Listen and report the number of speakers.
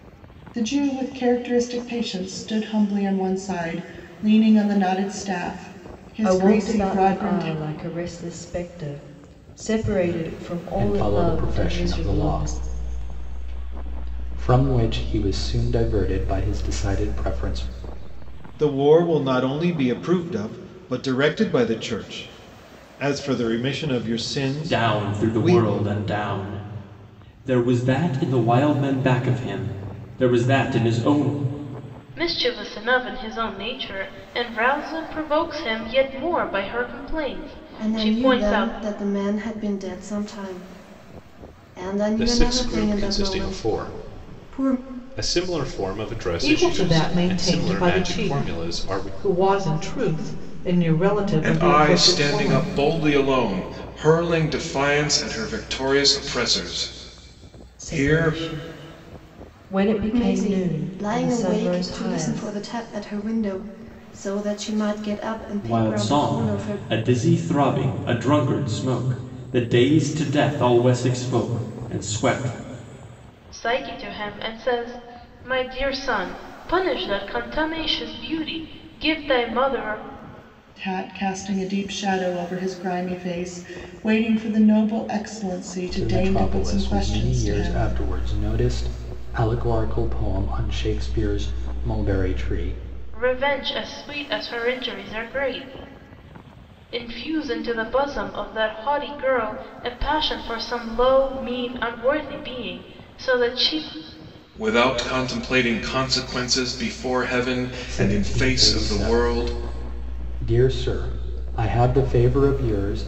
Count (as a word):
ten